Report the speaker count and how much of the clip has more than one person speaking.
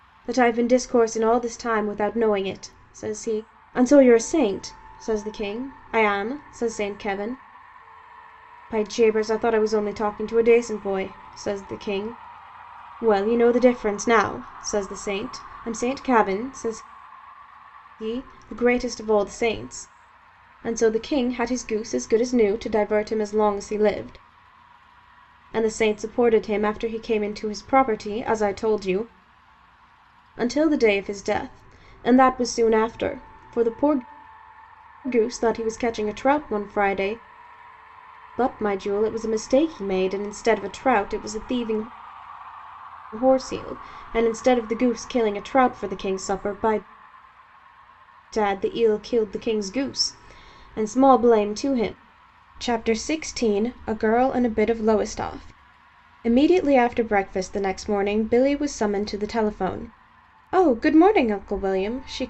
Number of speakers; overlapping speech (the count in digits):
1, no overlap